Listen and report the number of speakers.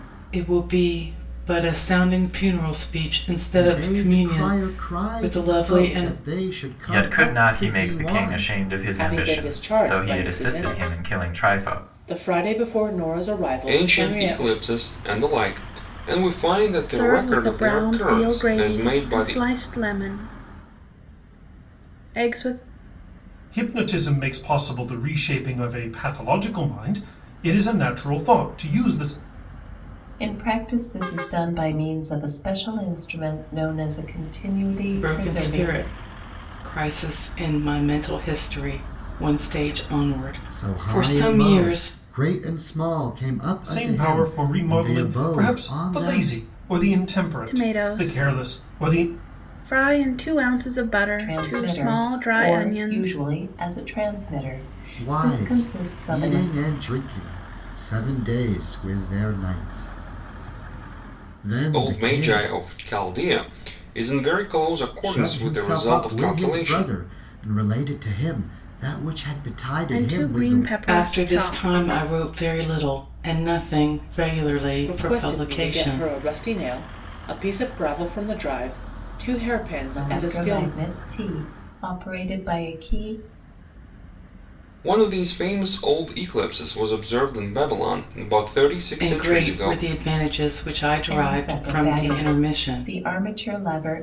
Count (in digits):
8